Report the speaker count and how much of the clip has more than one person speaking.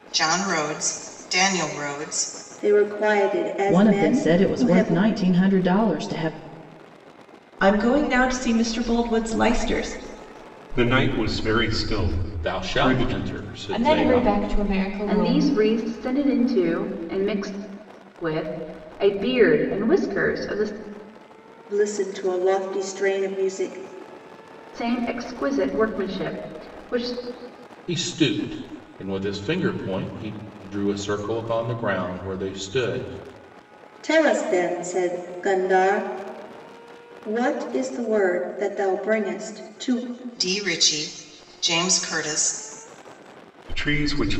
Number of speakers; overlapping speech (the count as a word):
eight, about 8%